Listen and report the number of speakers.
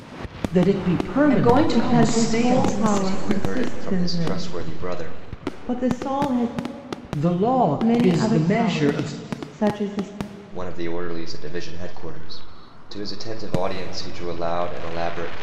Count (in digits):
4